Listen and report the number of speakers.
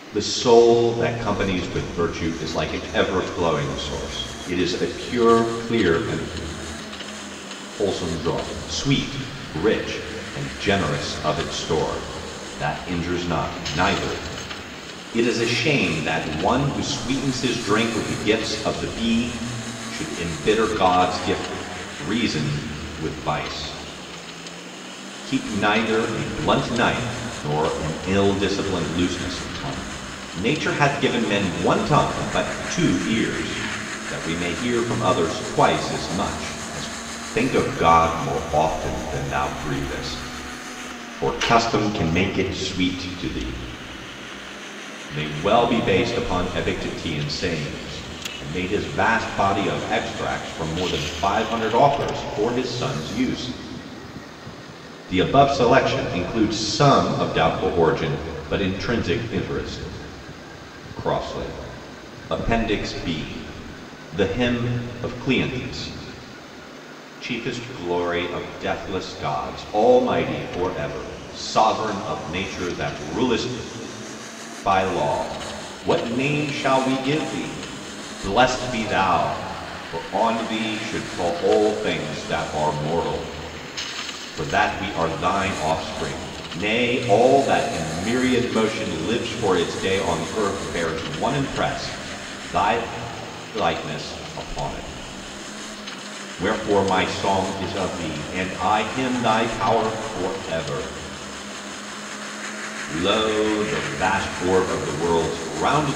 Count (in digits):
1